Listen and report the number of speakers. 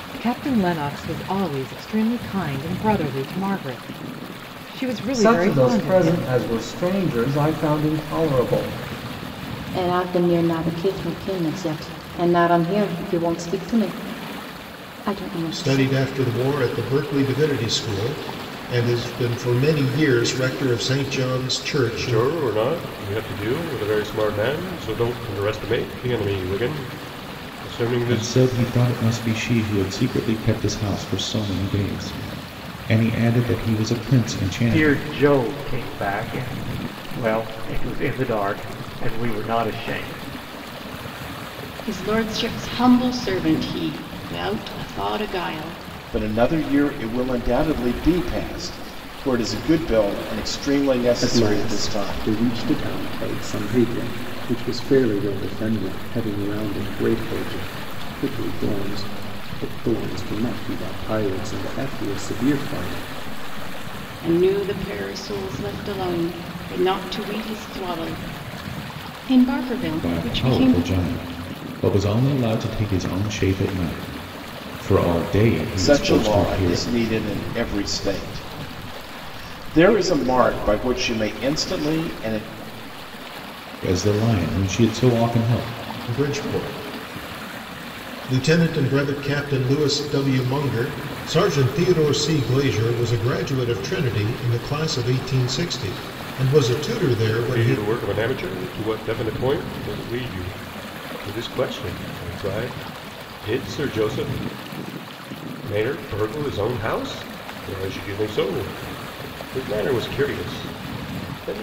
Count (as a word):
ten